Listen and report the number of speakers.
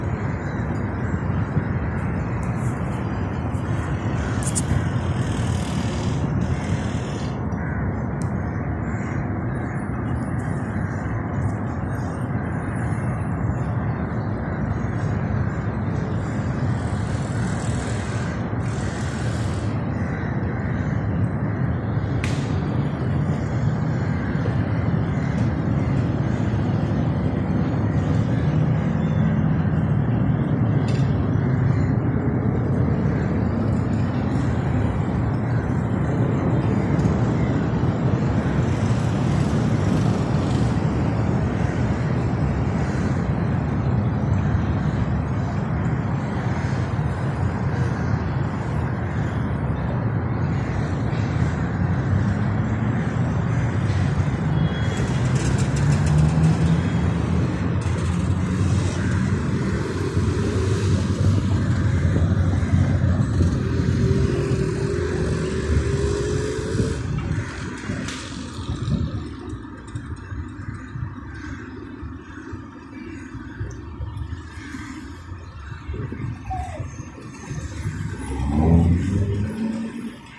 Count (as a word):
zero